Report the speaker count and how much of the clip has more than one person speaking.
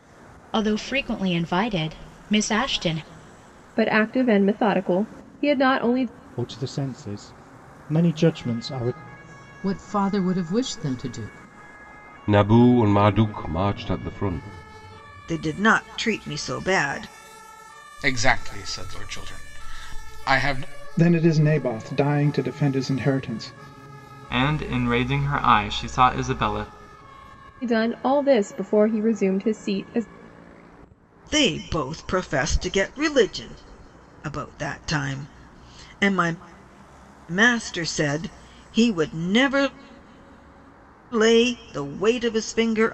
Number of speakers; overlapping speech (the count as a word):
nine, no overlap